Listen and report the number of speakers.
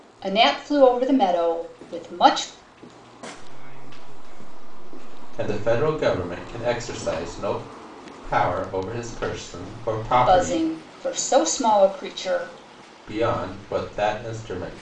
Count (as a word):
three